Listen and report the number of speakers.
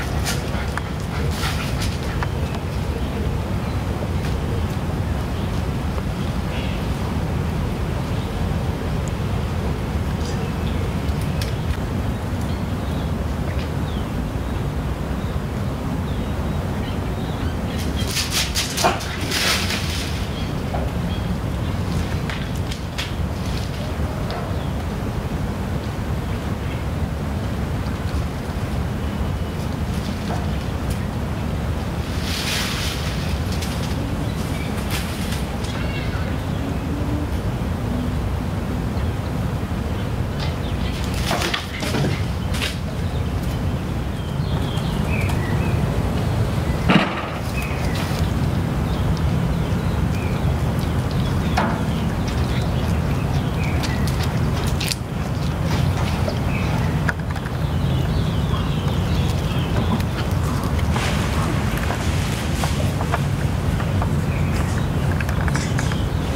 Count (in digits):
0